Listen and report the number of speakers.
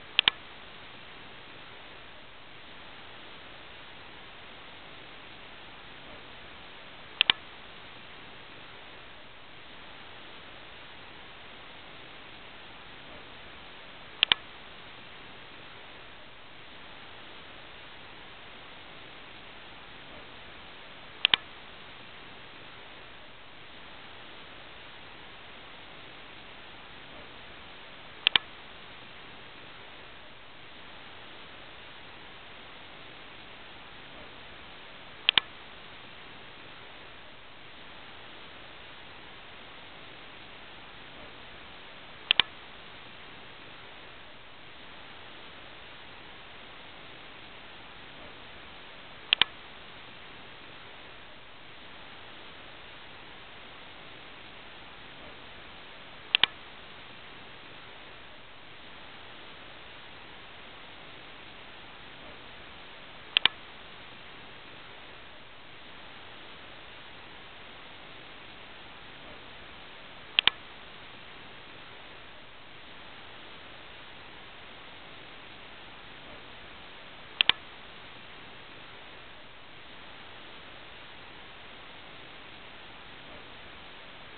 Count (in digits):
0